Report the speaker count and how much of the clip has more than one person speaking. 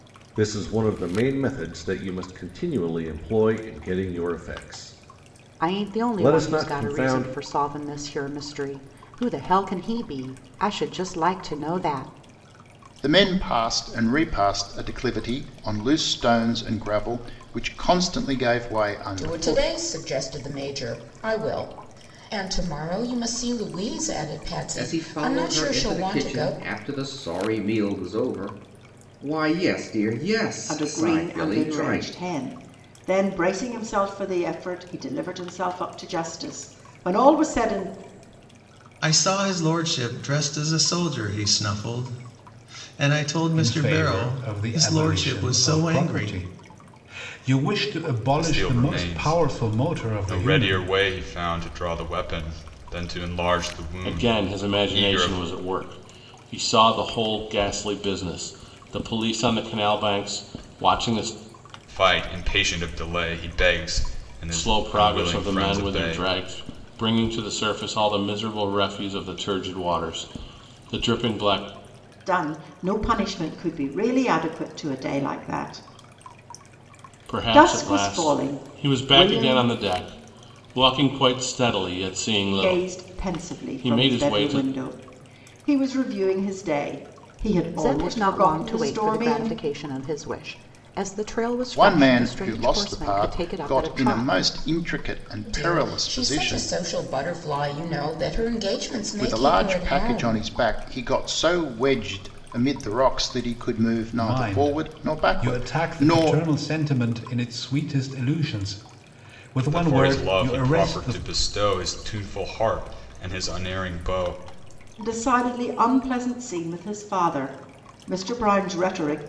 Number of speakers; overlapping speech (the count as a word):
ten, about 25%